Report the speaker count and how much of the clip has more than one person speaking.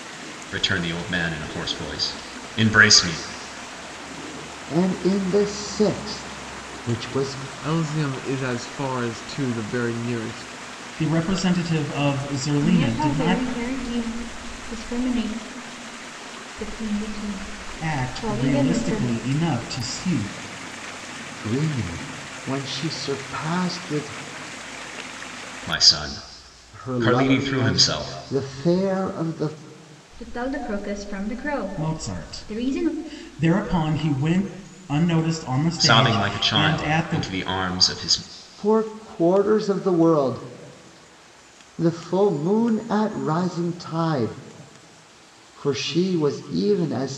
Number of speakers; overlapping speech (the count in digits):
5, about 13%